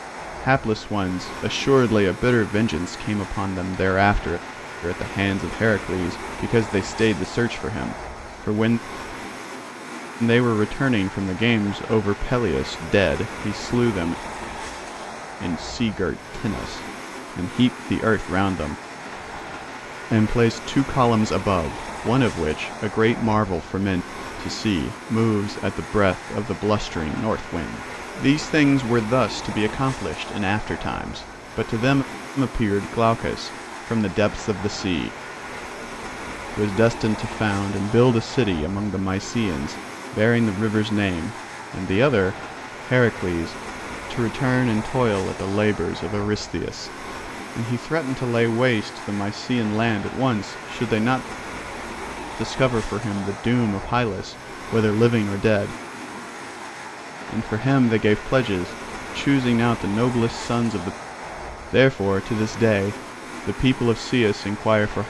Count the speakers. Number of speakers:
1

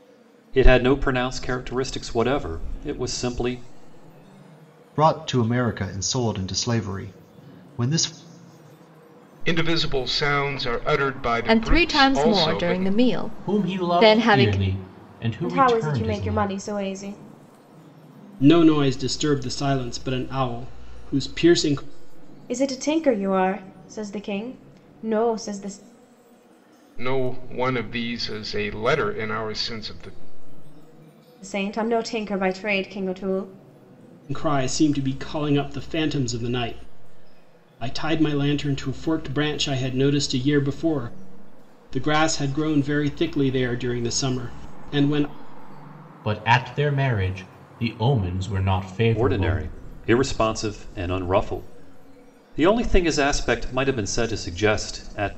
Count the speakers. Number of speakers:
7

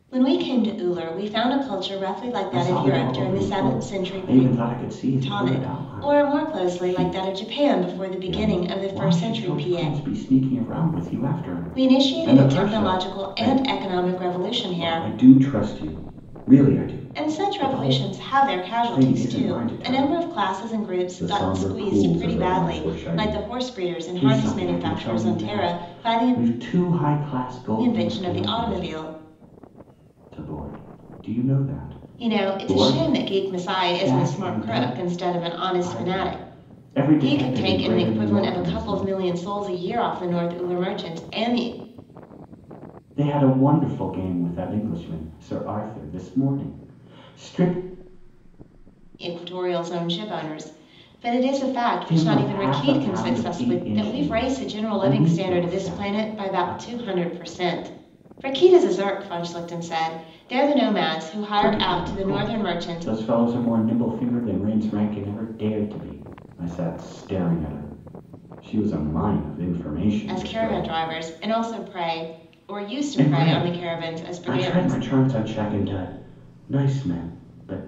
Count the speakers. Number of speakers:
2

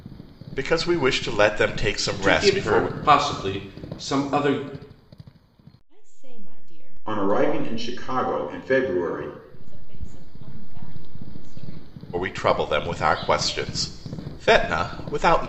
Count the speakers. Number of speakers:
4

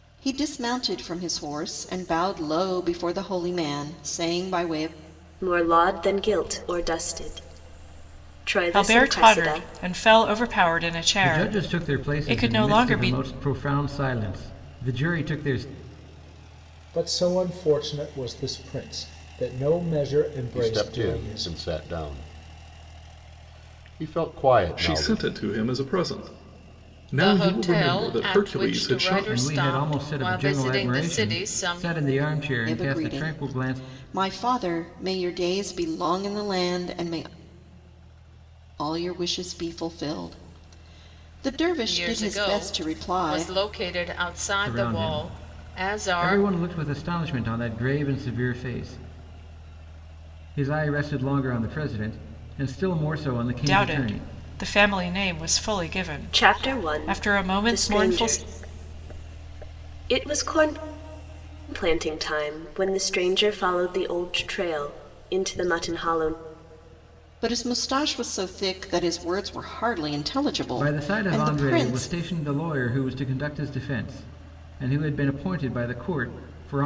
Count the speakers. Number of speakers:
8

